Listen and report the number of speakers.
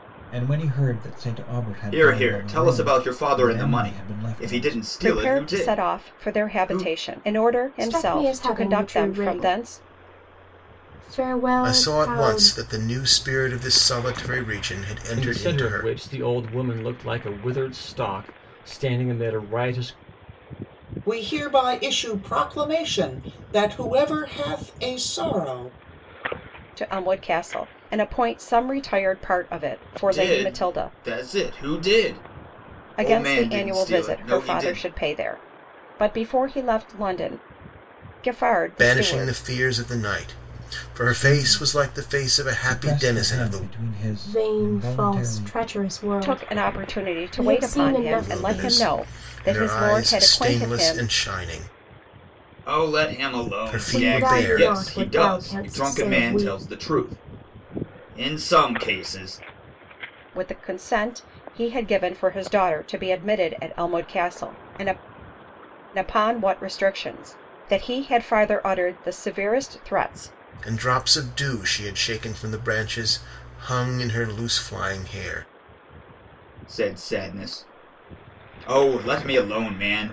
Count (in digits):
7